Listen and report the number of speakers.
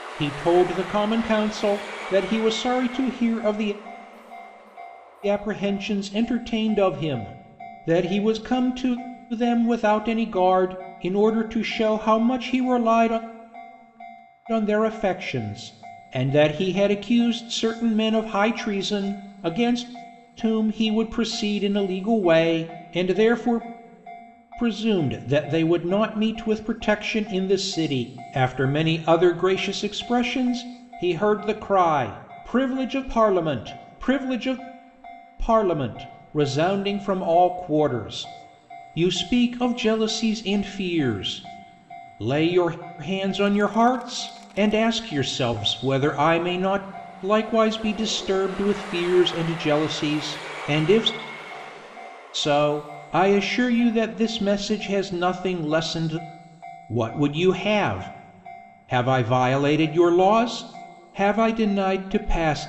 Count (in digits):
1